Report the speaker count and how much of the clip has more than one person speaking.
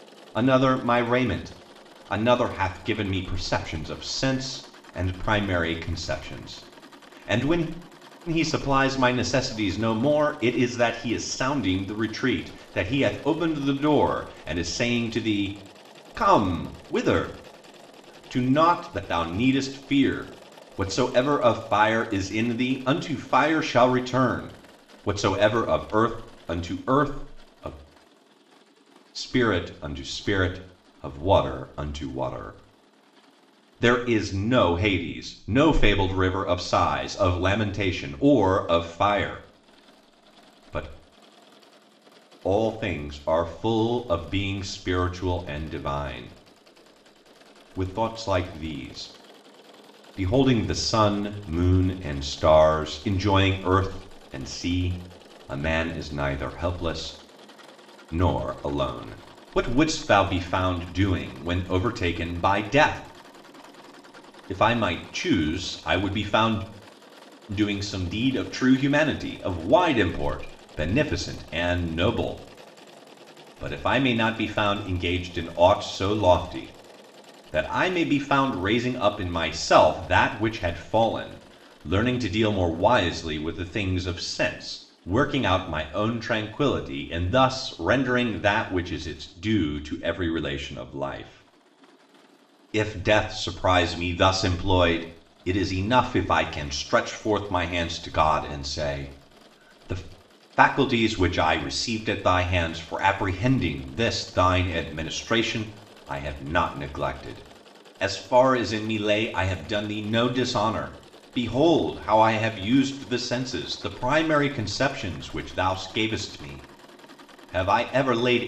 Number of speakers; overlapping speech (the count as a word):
one, no overlap